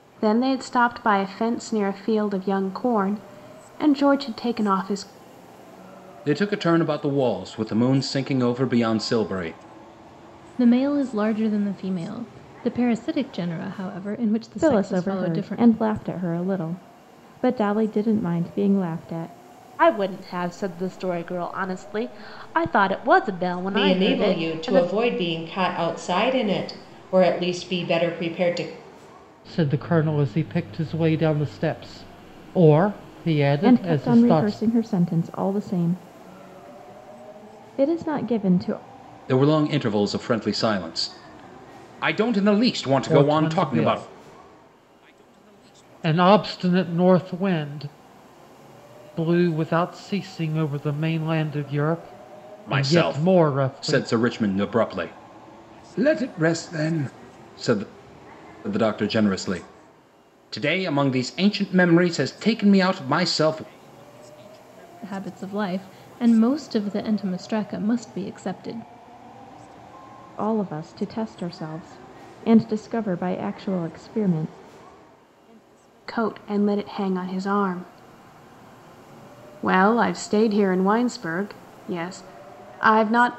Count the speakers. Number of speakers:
seven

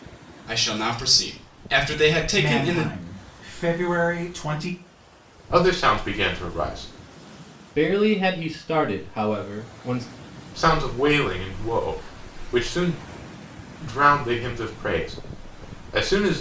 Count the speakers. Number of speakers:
four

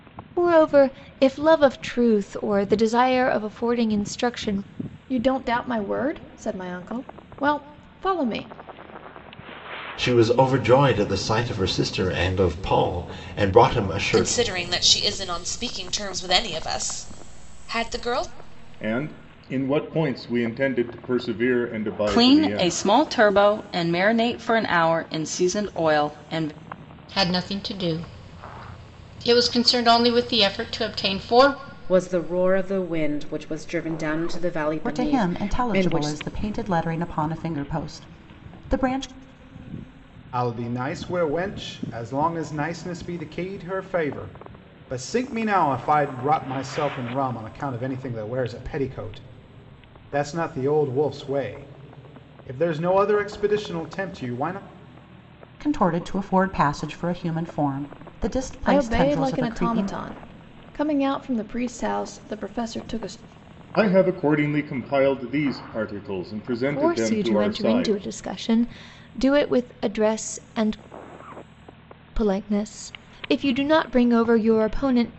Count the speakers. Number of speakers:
ten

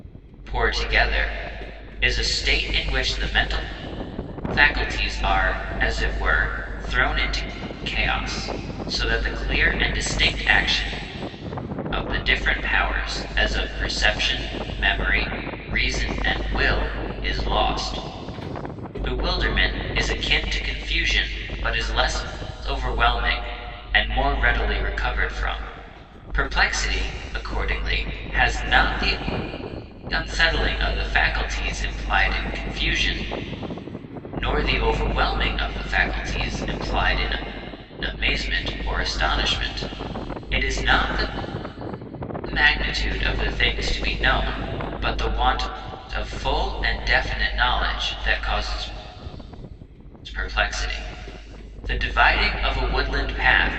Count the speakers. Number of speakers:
one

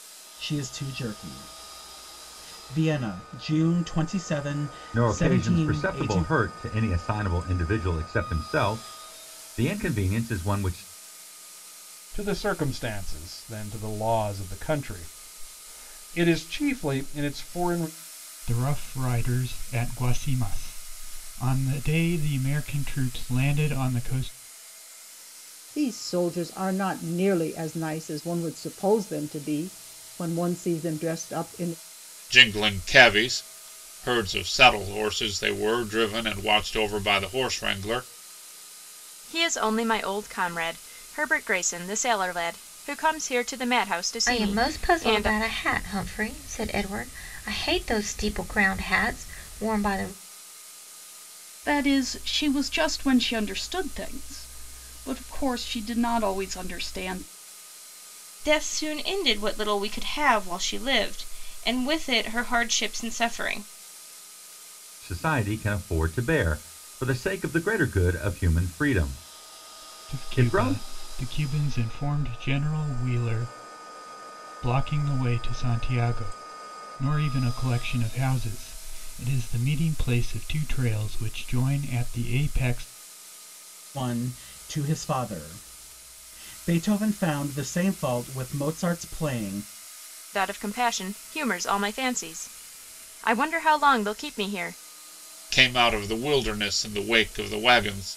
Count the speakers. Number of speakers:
ten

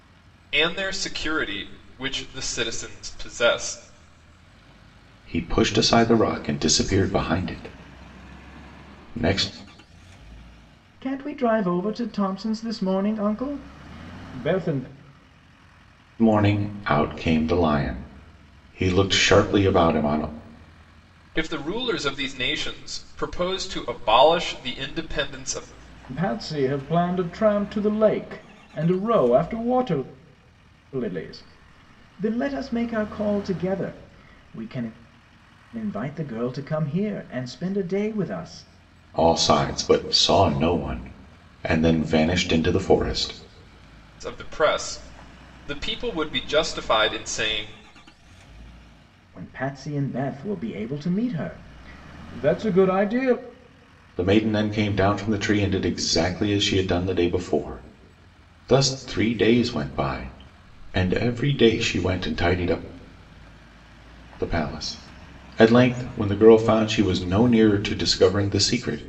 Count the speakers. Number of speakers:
three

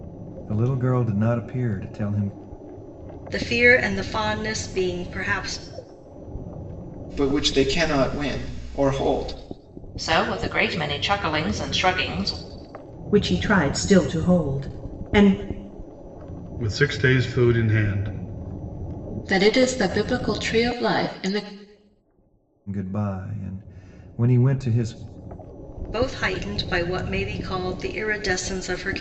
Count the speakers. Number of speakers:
seven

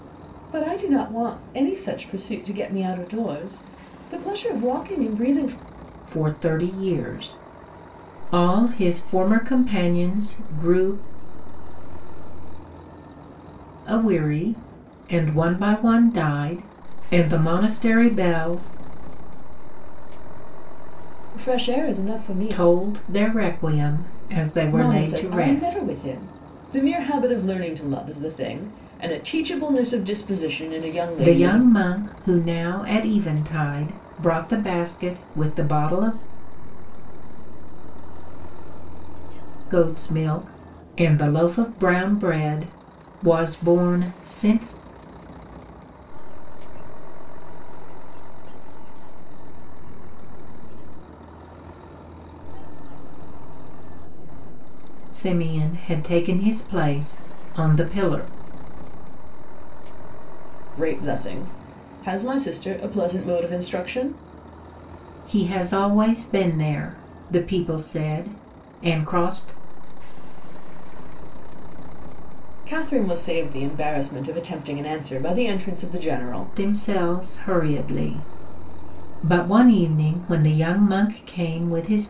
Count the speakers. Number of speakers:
three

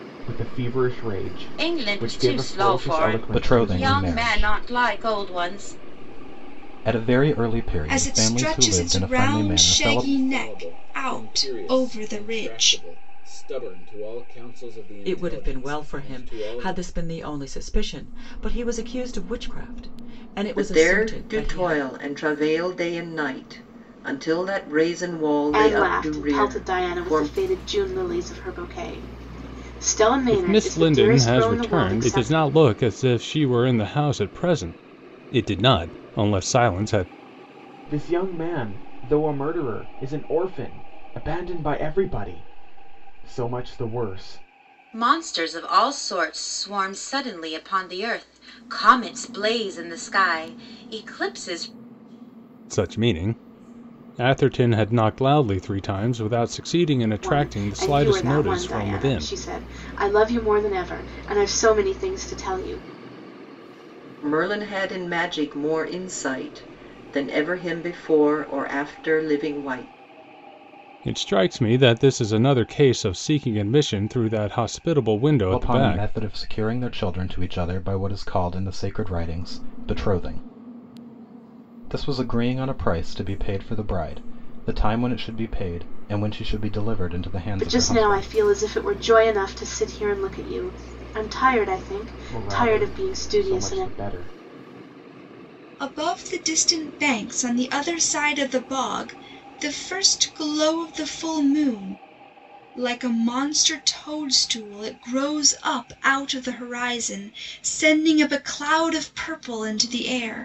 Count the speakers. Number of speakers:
nine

